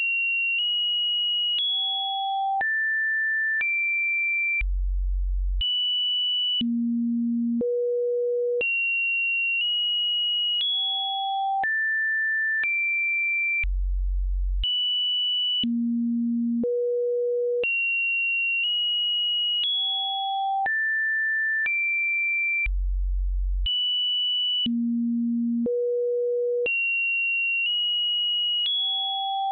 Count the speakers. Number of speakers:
zero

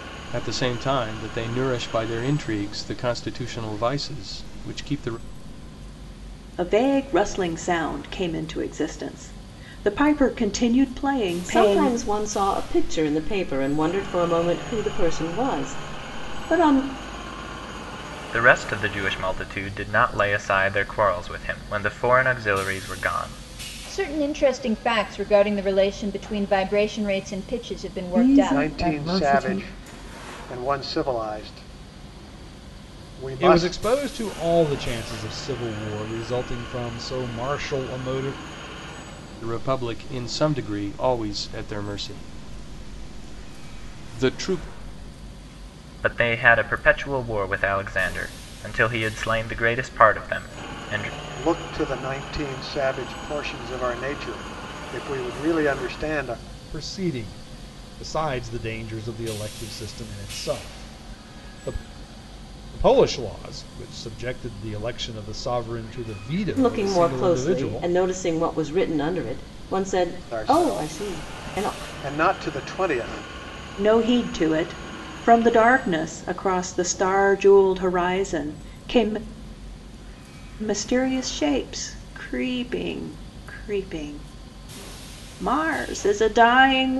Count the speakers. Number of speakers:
eight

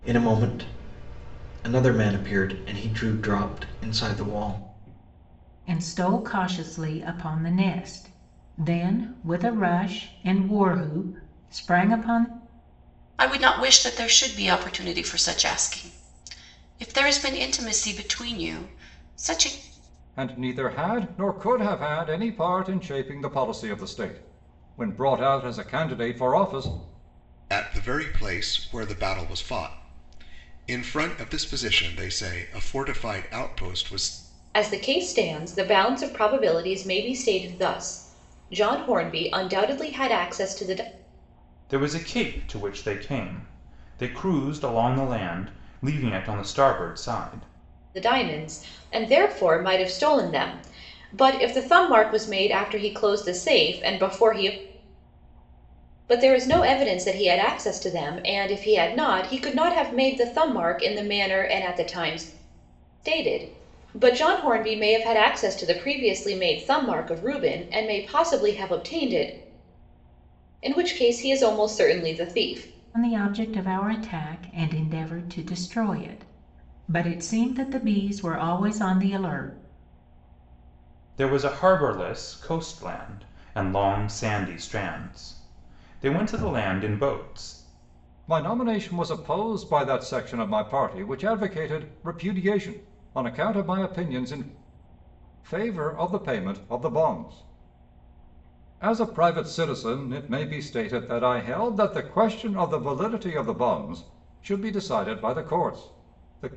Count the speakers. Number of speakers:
seven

